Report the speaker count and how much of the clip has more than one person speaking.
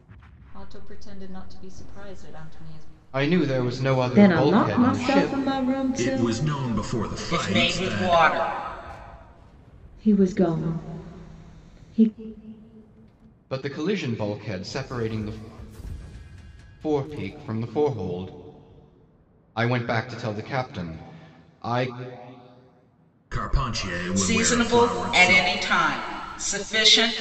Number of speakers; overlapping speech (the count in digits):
5, about 15%